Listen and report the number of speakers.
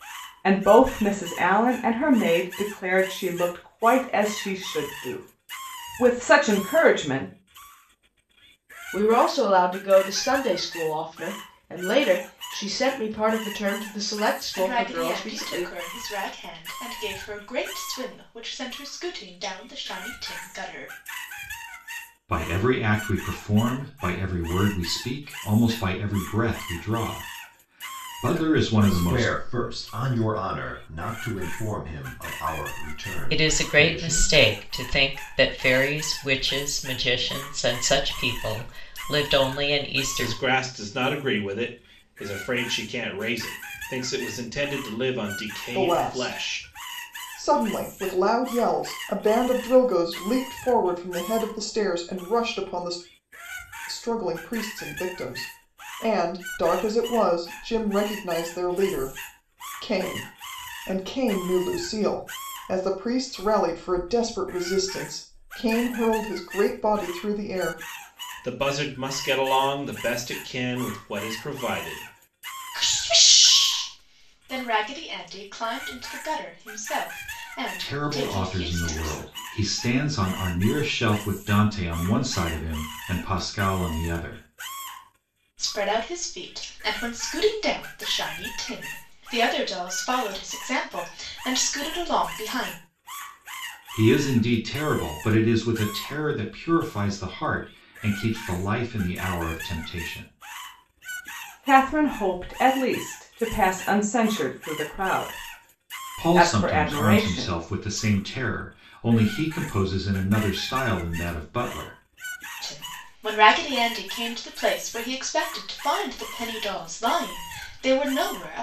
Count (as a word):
eight